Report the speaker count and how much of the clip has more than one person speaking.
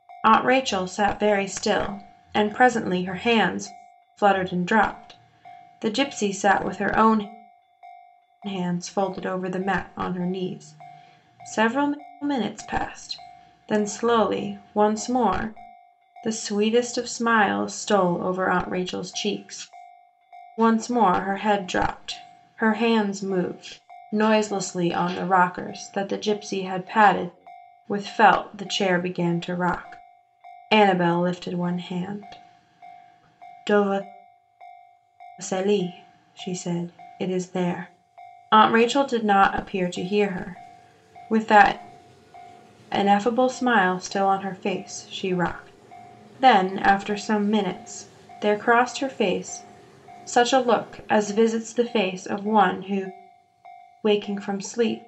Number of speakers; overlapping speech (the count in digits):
1, no overlap